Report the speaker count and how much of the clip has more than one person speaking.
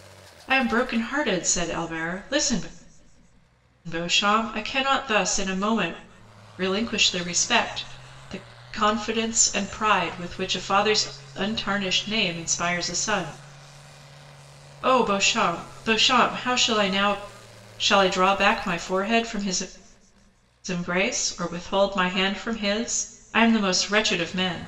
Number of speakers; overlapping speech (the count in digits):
1, no overlap